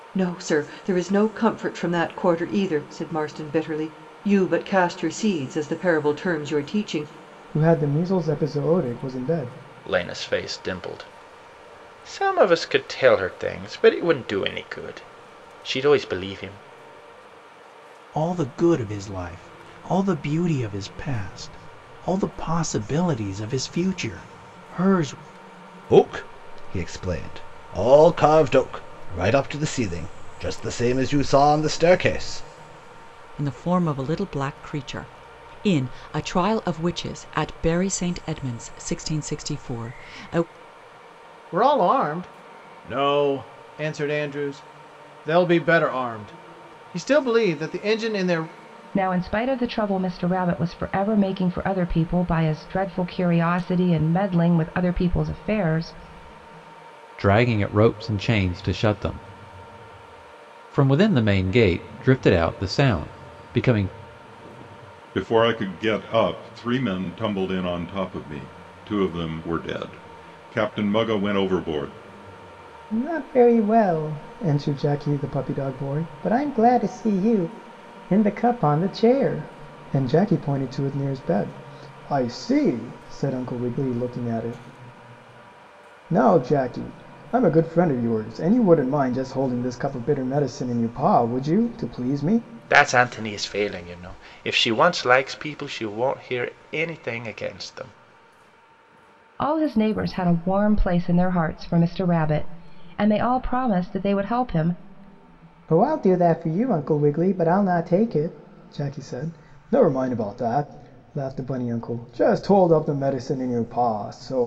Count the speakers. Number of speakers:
10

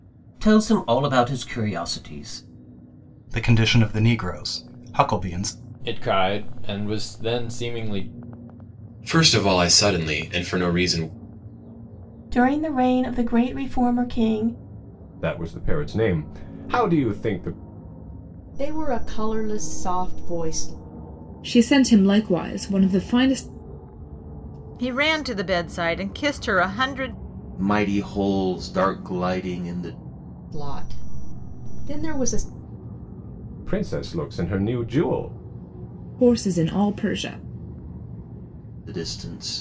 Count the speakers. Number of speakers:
10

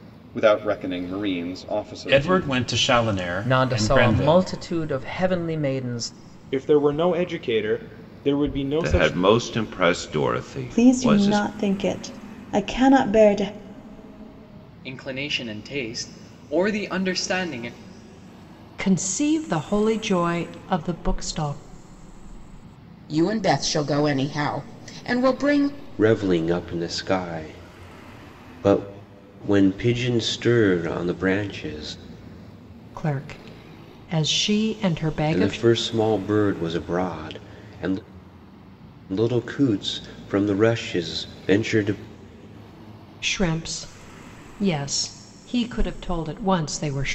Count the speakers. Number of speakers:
10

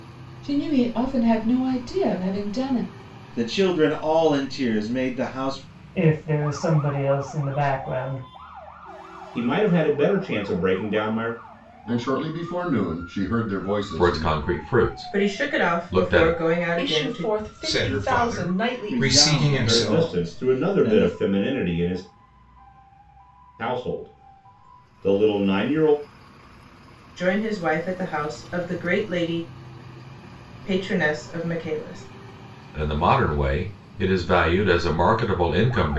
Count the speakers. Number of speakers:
9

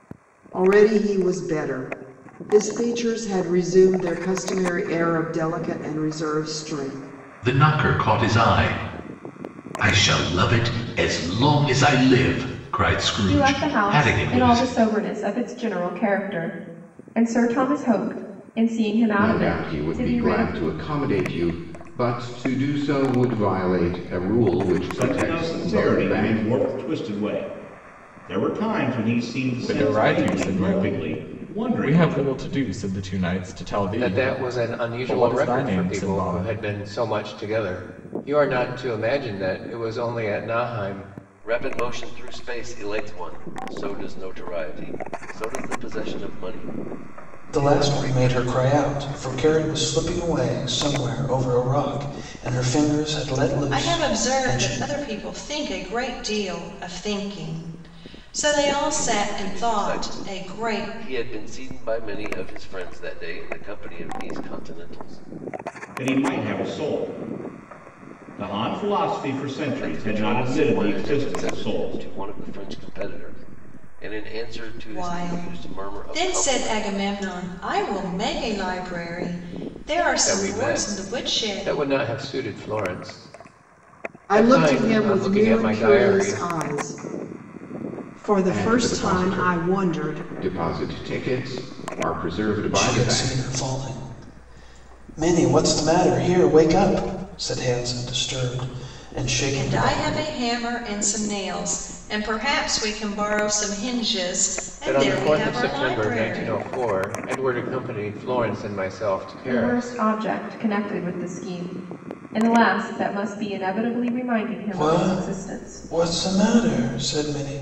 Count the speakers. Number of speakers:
10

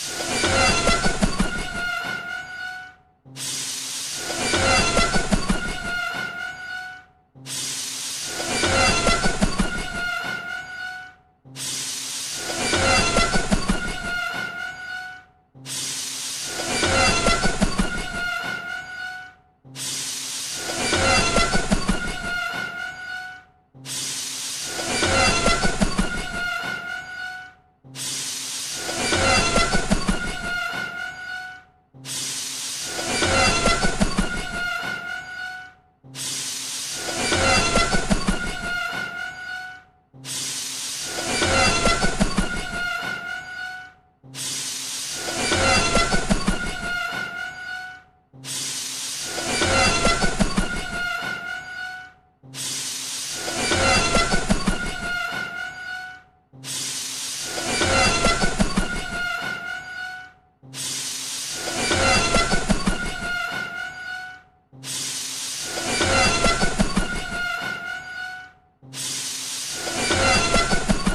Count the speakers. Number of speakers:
0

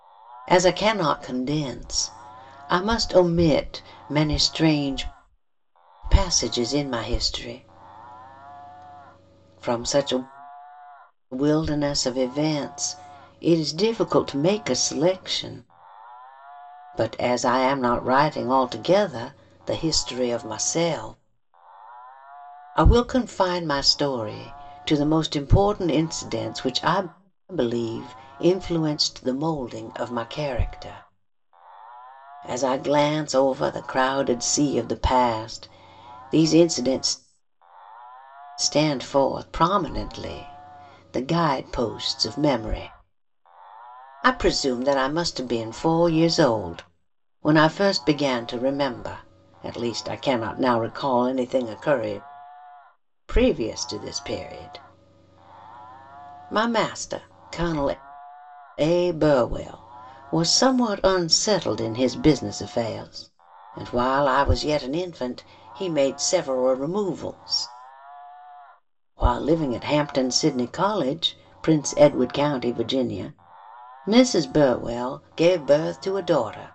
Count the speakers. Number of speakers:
1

